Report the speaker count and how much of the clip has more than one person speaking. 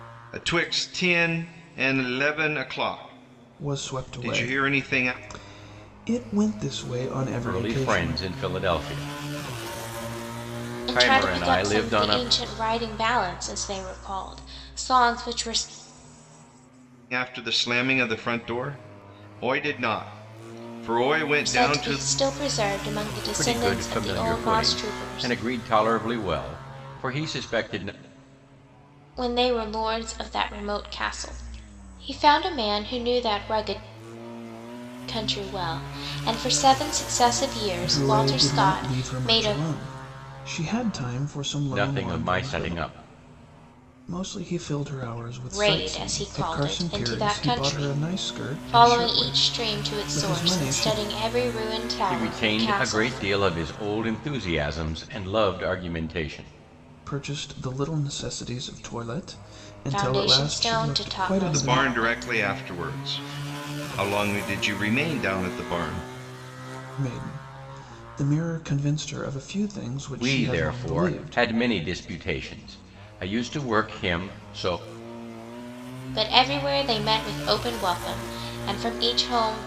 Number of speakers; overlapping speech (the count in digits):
4, about 24%